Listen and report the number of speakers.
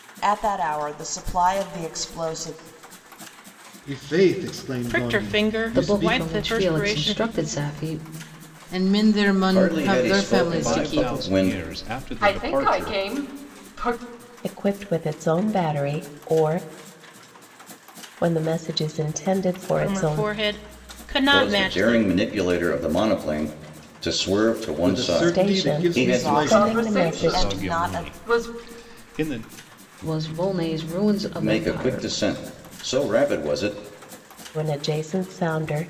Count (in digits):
9